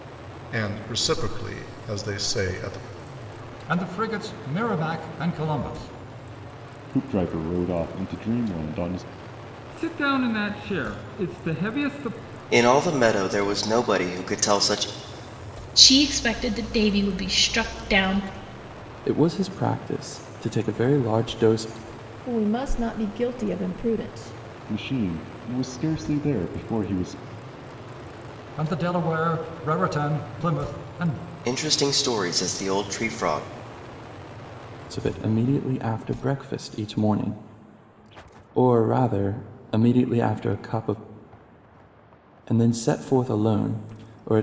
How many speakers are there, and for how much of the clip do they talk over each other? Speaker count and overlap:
eight, no overlap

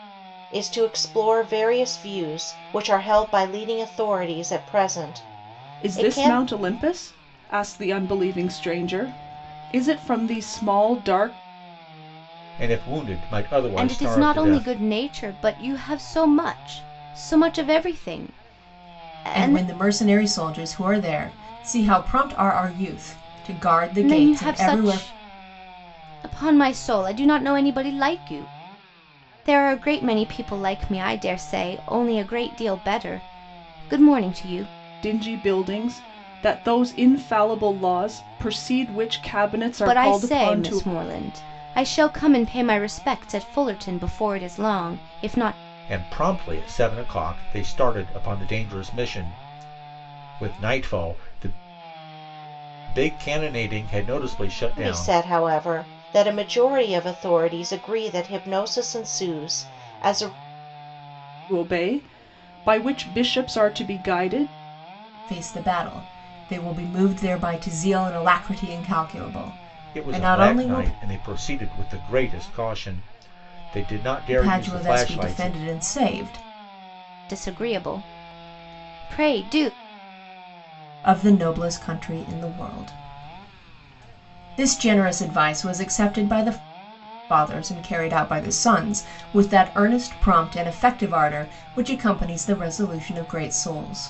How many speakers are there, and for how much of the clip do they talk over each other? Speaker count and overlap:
five, about 7%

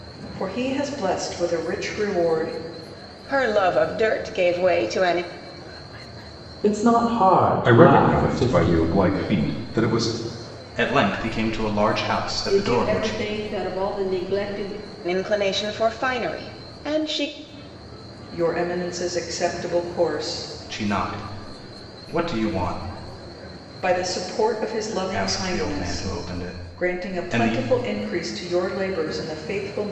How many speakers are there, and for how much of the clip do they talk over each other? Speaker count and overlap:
six, about 12%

